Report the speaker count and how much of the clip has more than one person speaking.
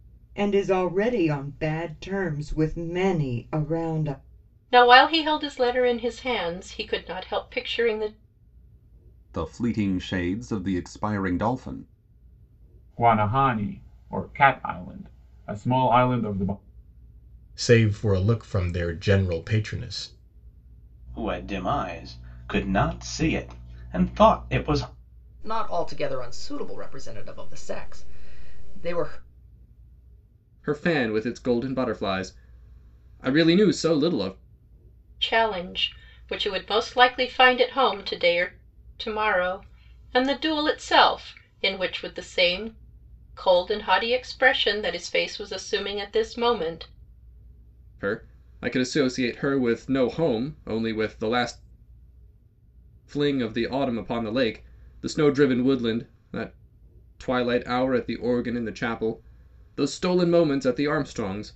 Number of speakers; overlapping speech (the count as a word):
eight, no overlap